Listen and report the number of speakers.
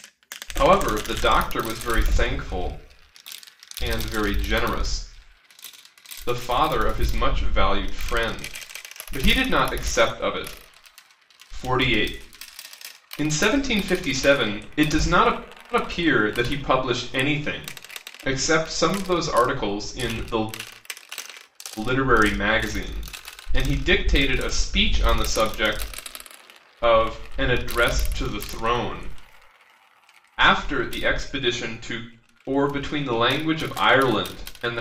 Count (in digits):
1